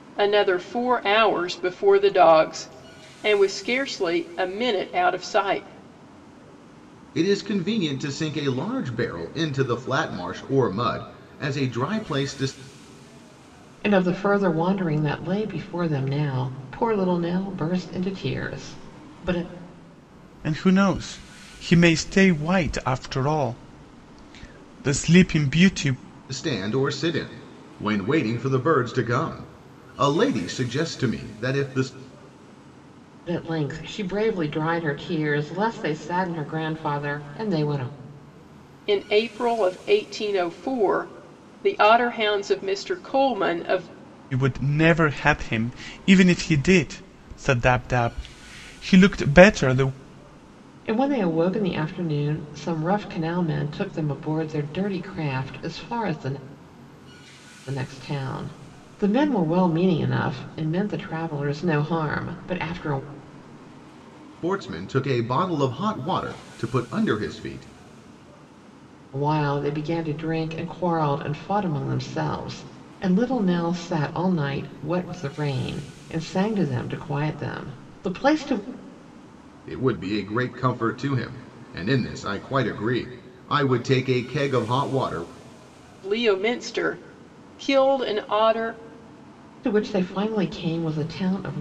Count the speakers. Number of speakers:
4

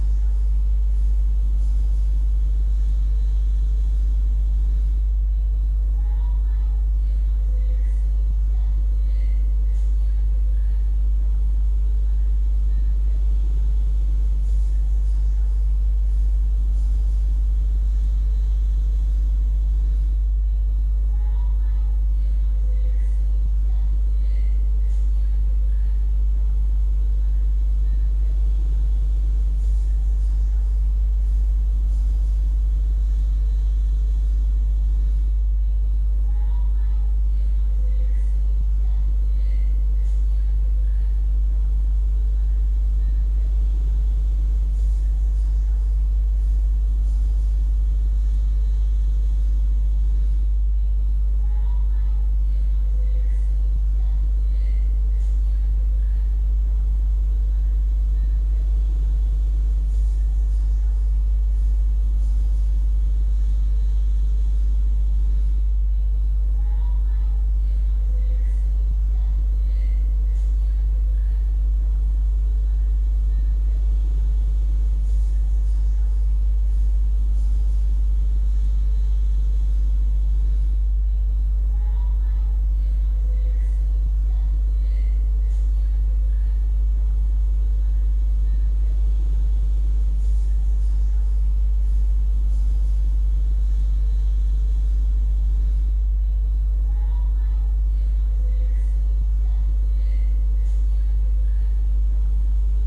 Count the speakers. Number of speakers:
0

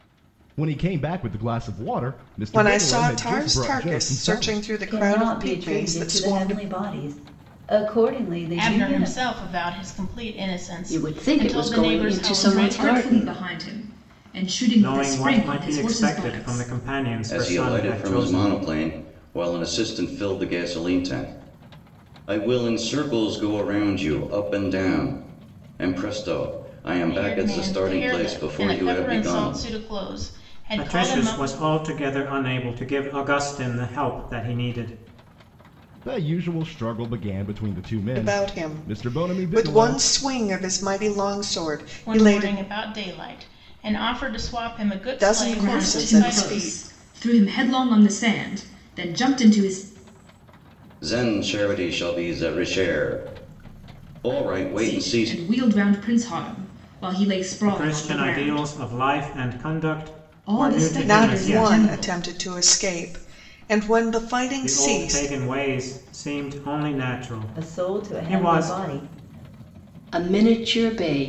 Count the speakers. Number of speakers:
8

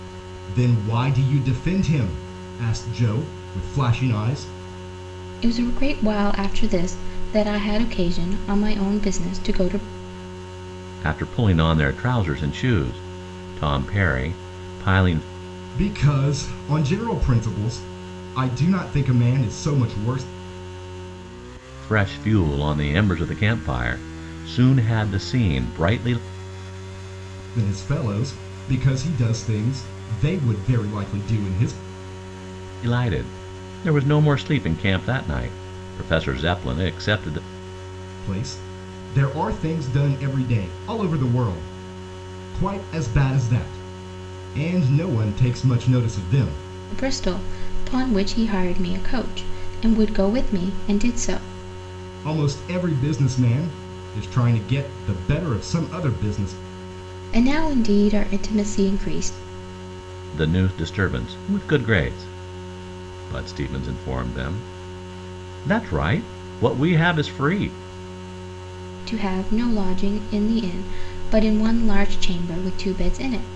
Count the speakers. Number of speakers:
3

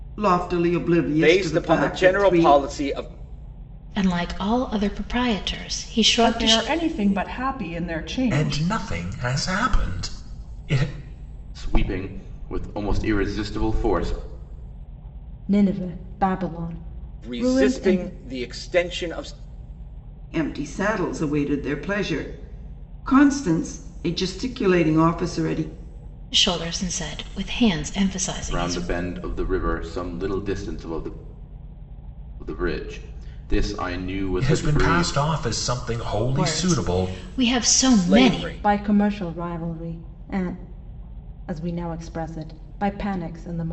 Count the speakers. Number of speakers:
7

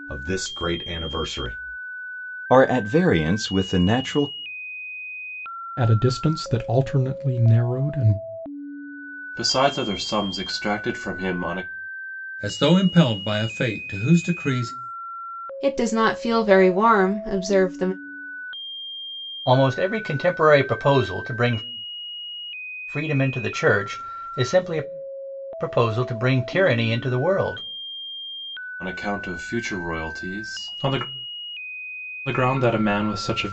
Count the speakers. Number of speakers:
7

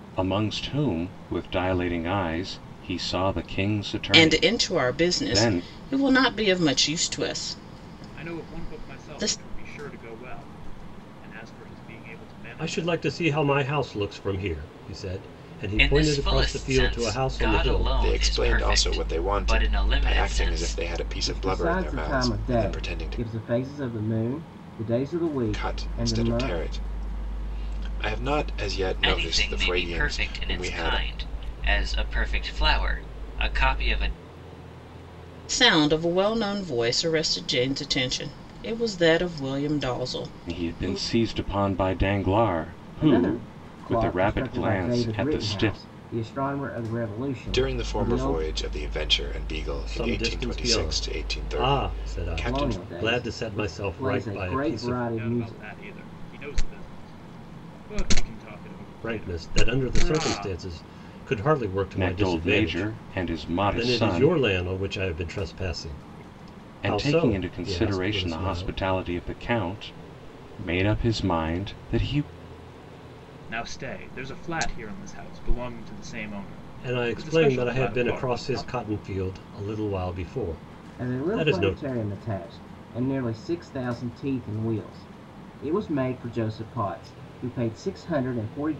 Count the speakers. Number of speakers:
7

